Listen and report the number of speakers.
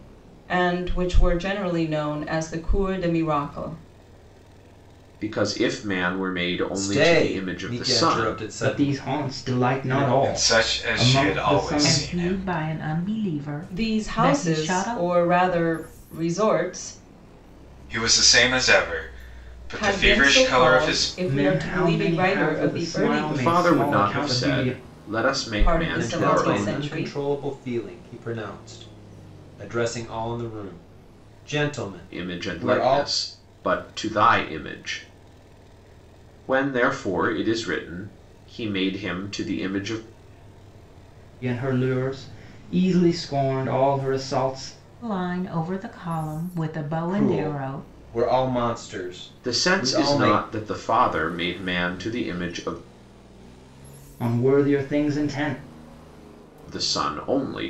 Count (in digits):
6